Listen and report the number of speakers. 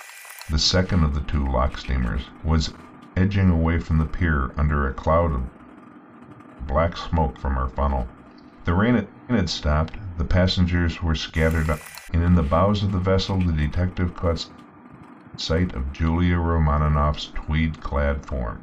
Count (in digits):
1